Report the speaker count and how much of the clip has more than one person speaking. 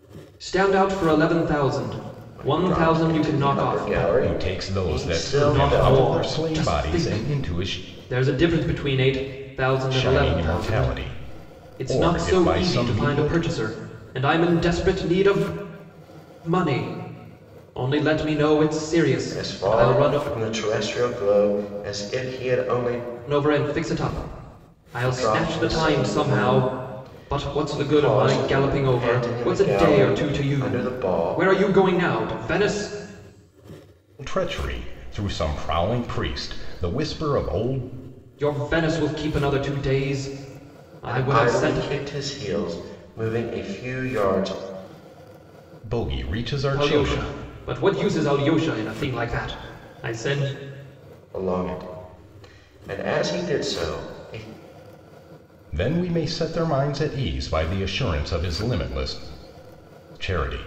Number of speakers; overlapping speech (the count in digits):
3, about 27%